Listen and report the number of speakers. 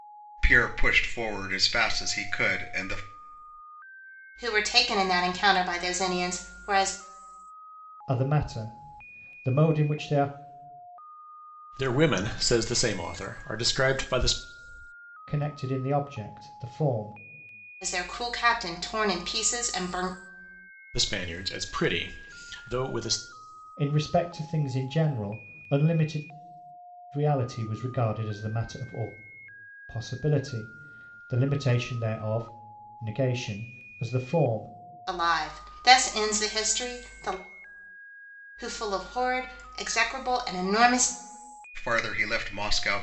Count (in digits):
4